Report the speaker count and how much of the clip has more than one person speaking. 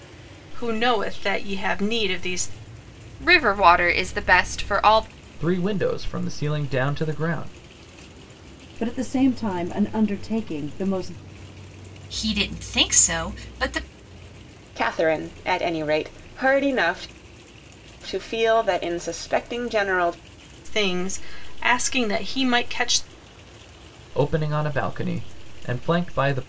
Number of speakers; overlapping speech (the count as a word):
six, no overlap